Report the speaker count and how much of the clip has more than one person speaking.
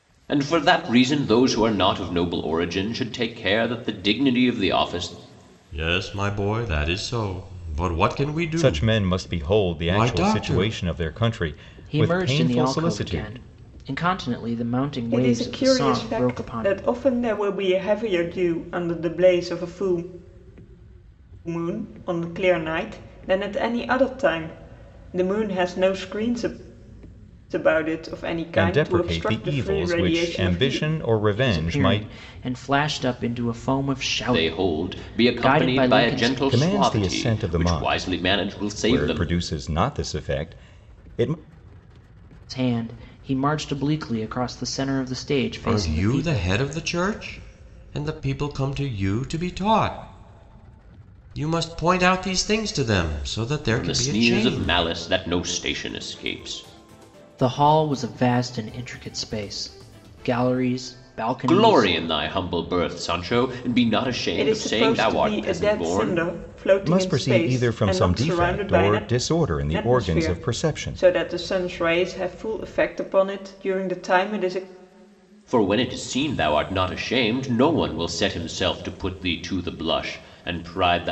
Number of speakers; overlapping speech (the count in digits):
5, about 27%